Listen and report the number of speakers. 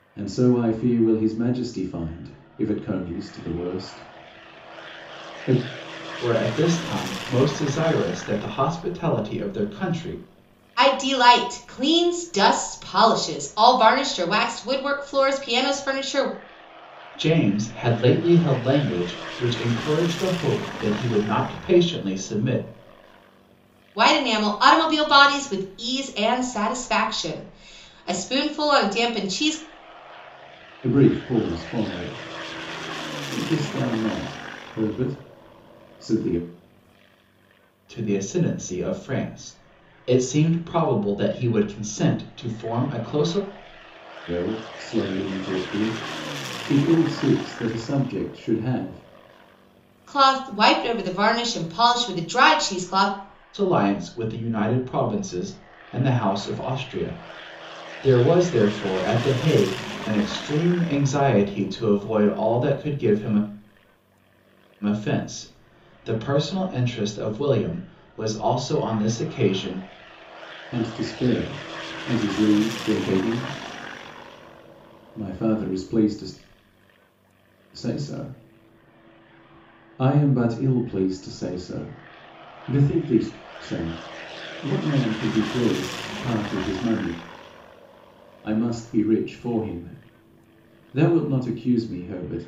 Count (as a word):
three